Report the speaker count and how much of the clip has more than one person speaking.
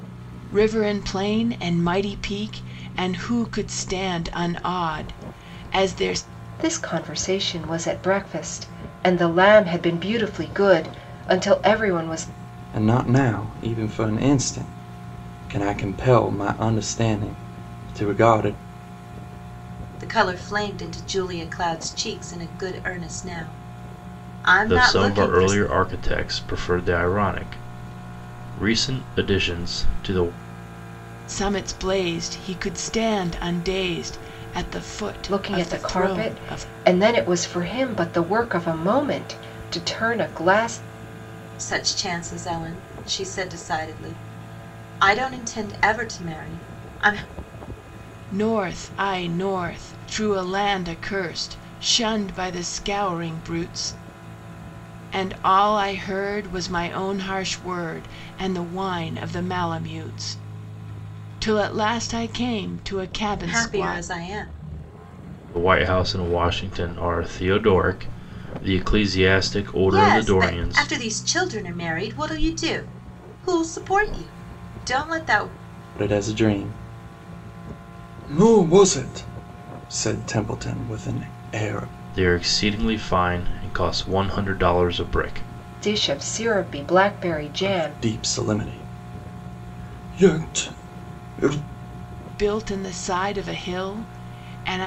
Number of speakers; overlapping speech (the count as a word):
five, about 5%